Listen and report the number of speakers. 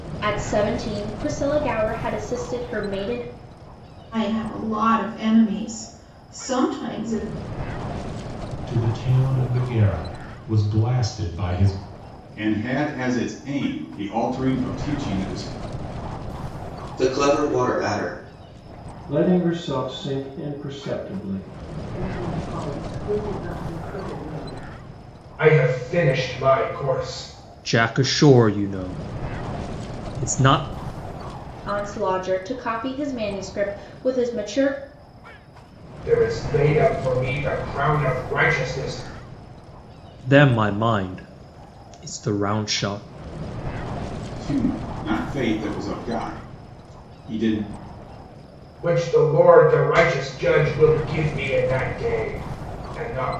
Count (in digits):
9